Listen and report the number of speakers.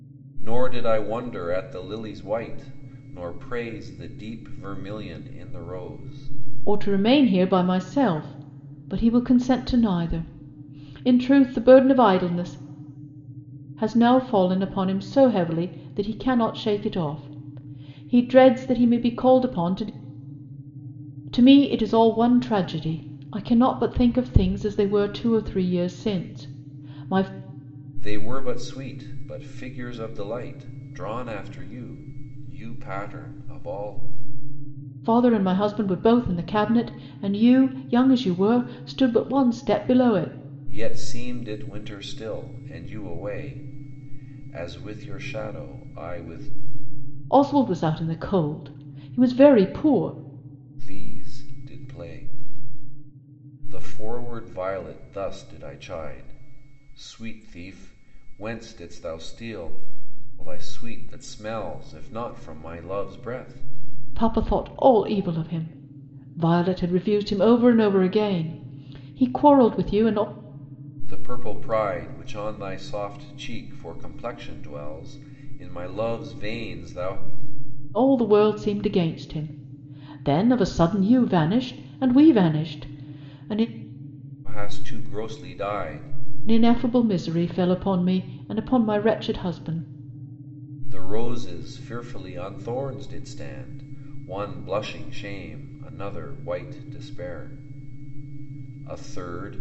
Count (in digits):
2